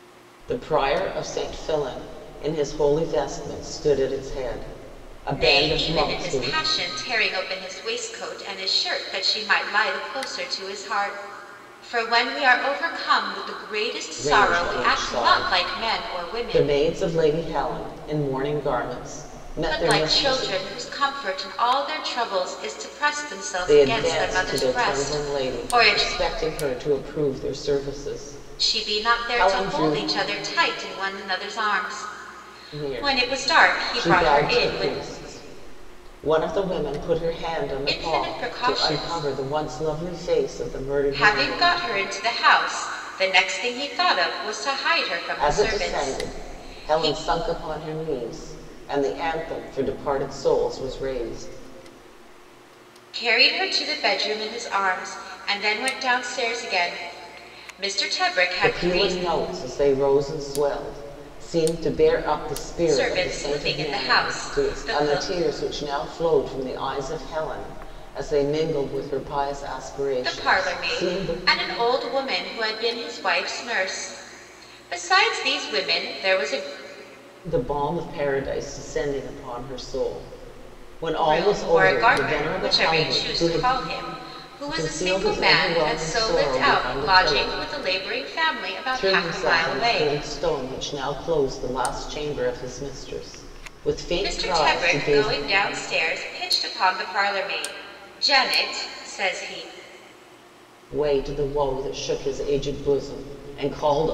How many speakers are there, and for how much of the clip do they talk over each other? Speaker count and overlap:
2, about 26%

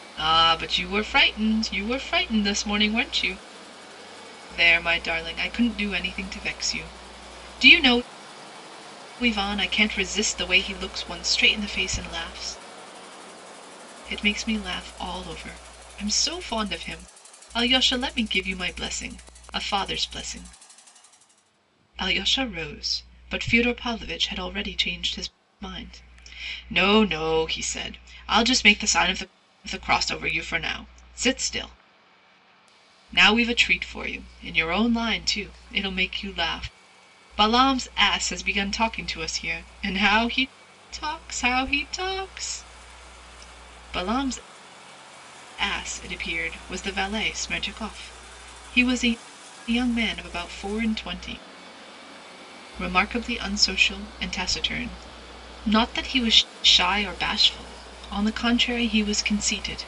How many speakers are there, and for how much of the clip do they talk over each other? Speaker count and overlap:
1, no overlap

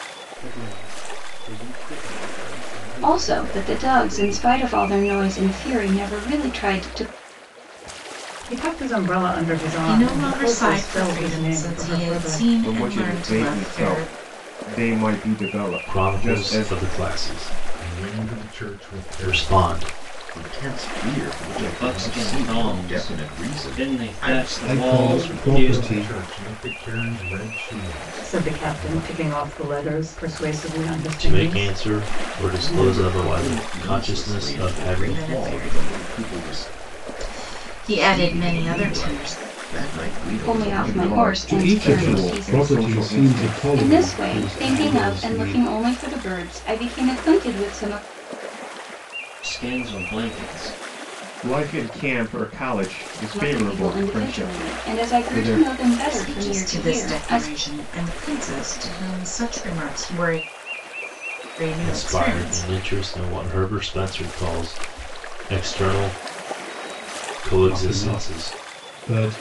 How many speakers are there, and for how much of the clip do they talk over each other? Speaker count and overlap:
10, about 47%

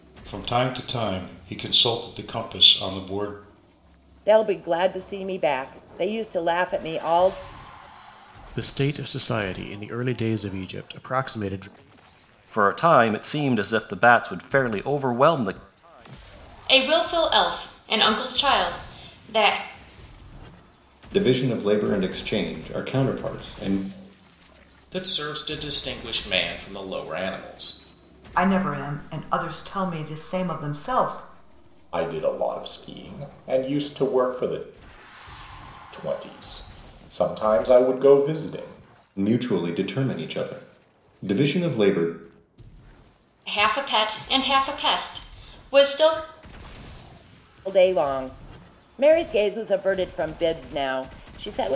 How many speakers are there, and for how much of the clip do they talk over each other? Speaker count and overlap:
9, no overlap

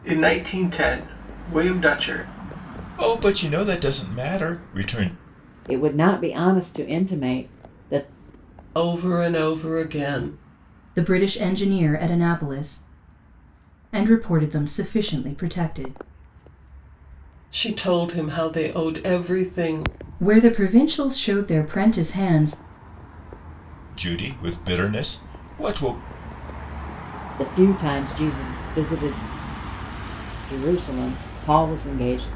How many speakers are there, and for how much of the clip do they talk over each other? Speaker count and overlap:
5, no overlap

